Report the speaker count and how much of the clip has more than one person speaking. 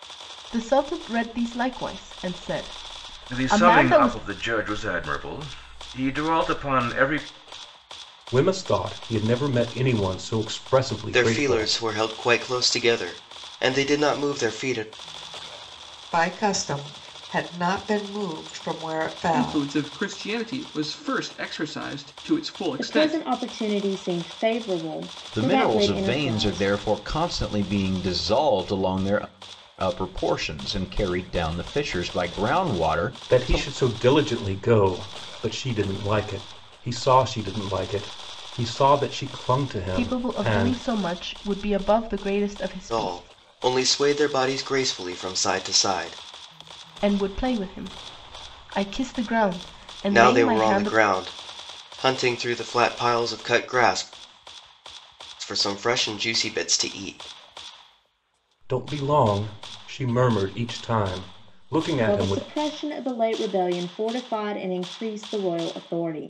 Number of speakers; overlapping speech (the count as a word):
eight, about 11%